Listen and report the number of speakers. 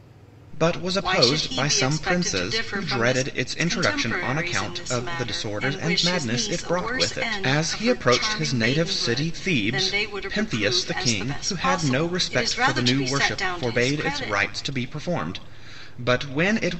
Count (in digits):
2